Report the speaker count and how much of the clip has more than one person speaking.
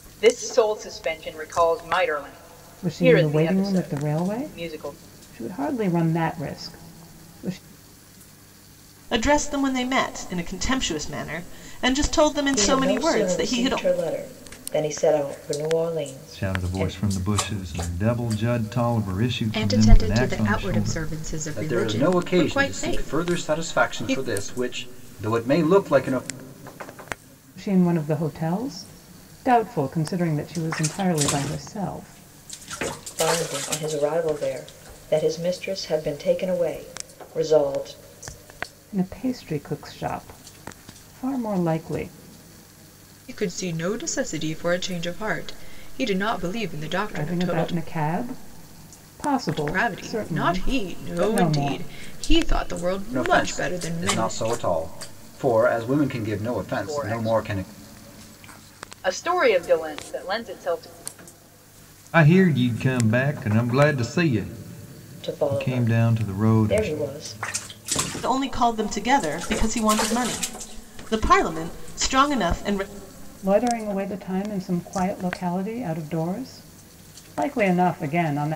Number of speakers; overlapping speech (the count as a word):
seven, about 20%